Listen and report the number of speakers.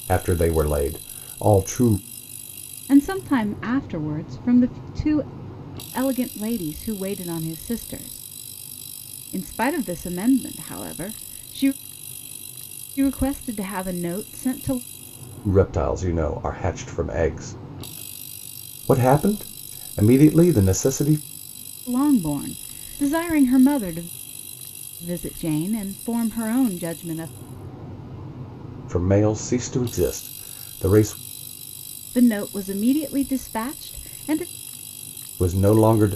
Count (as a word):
two